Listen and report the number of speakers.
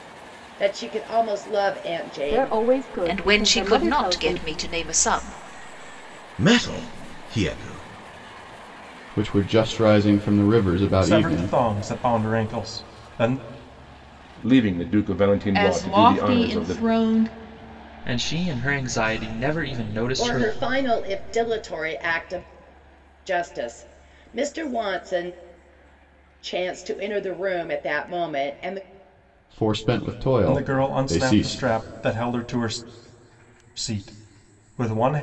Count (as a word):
nine